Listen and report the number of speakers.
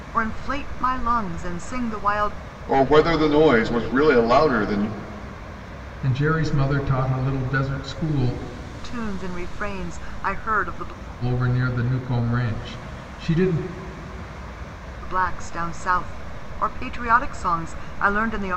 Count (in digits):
3